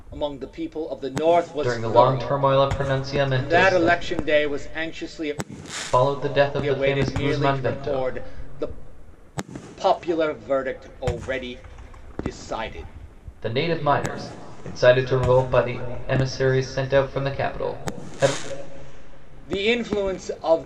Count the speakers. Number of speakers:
2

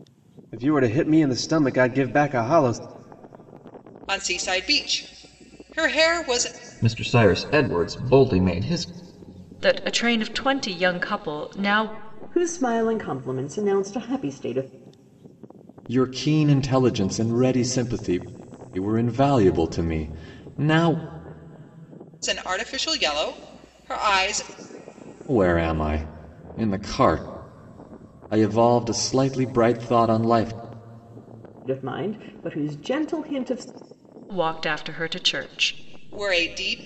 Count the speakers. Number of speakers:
6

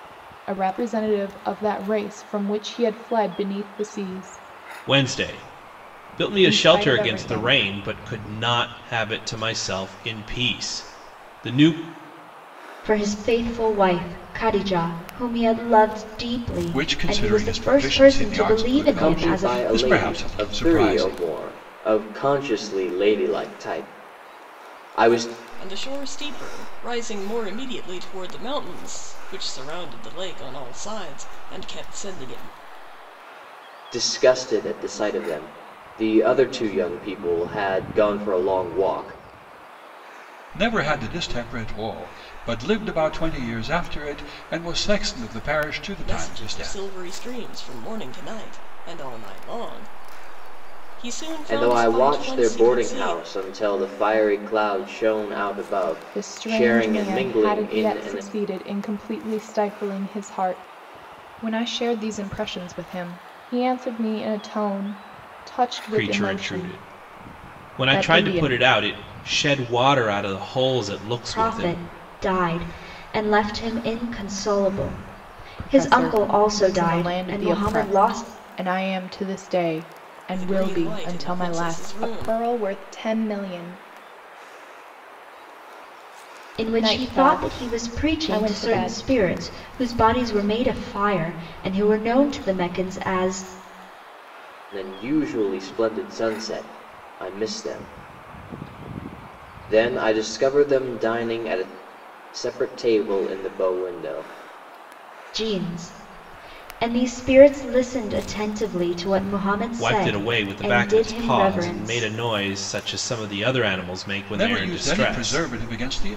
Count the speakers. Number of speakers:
6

